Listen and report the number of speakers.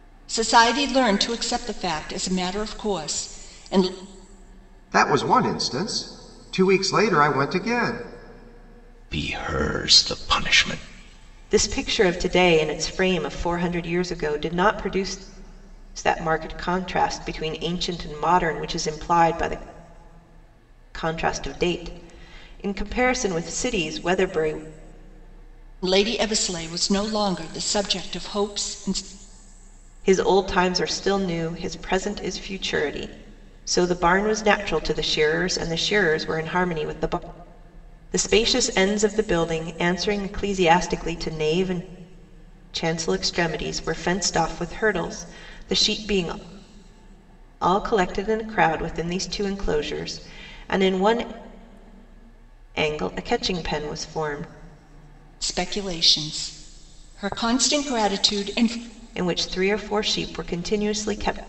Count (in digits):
4